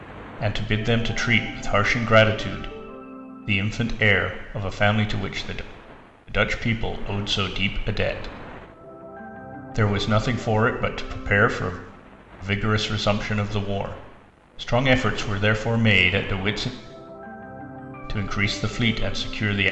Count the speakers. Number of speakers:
1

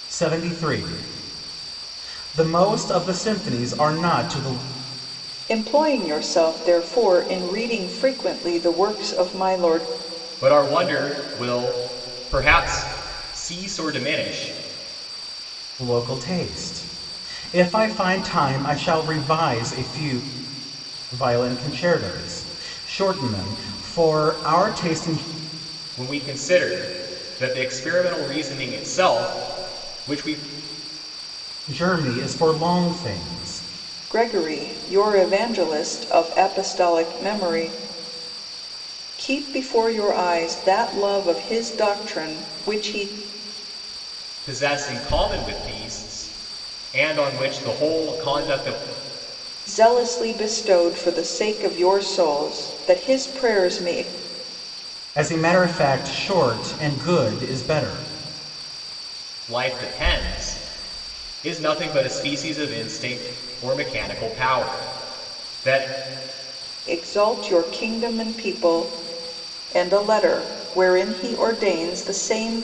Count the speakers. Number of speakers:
3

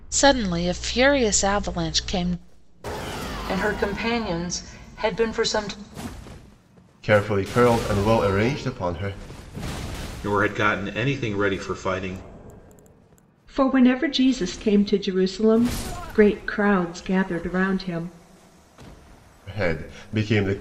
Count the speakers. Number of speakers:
5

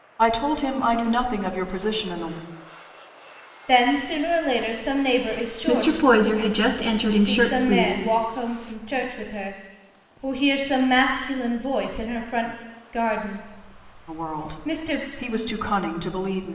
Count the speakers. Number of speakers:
3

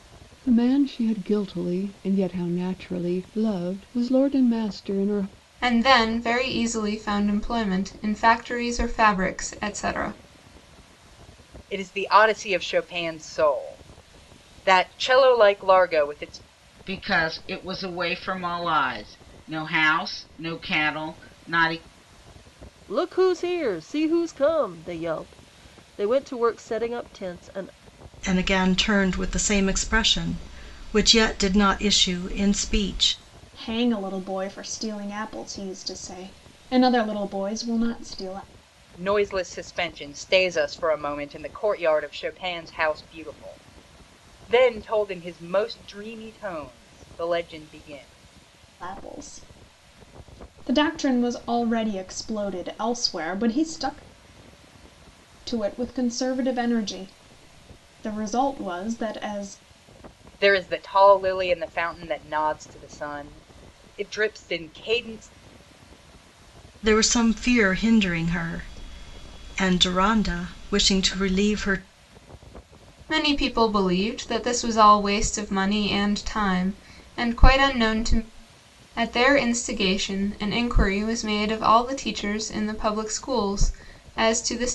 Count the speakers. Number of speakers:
7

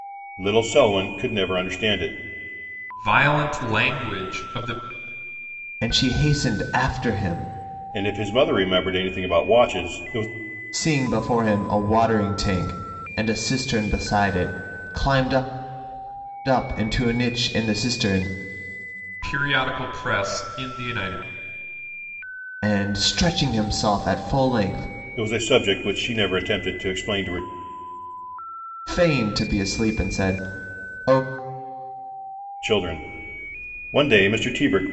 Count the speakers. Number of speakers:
3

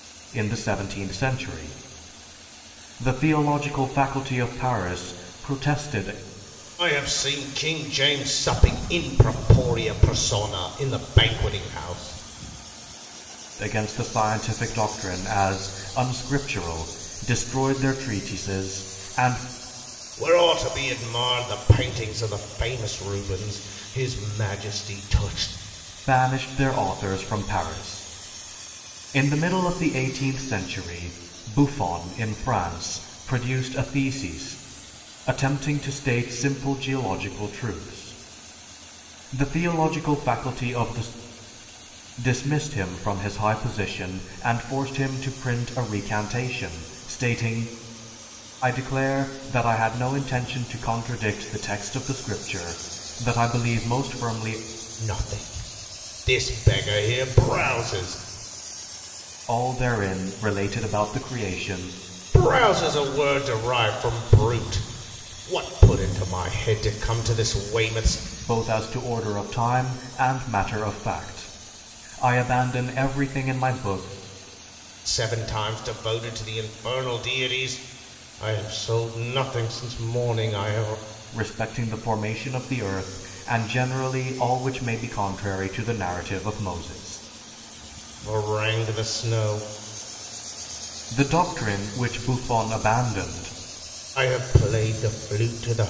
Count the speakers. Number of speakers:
2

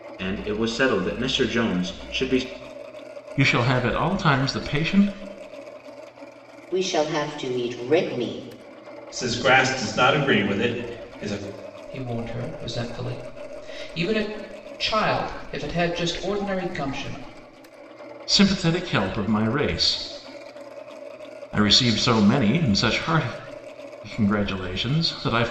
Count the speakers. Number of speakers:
5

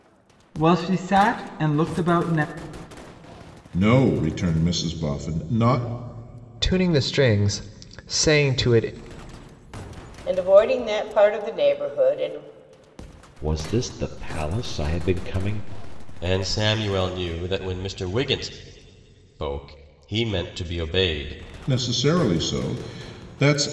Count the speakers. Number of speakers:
6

